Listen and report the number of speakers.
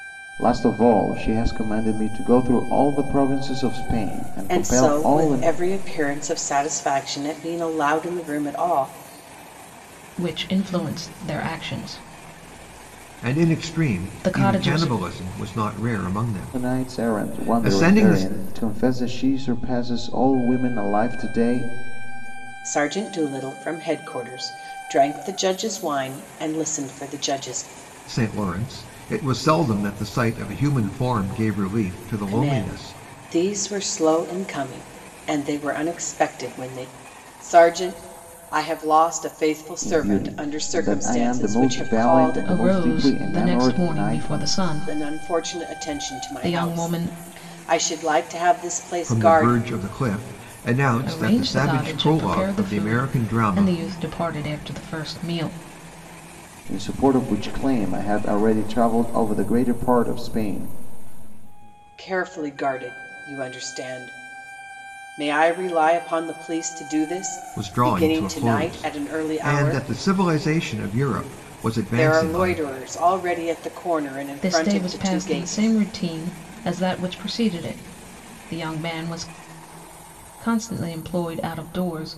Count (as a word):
four